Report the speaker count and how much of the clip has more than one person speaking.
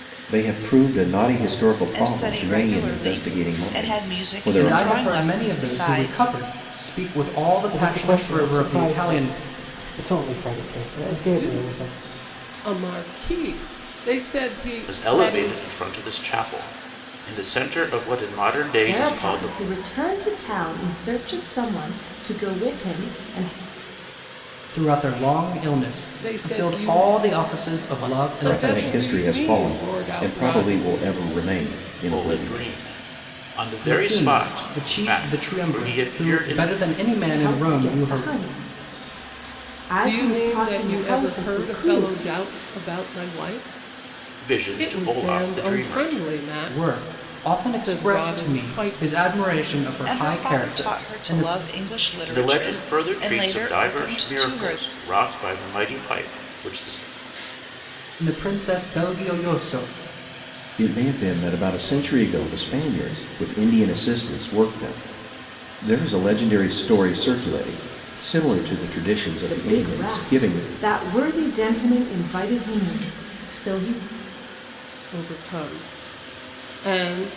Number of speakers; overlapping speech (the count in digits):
7, about 38%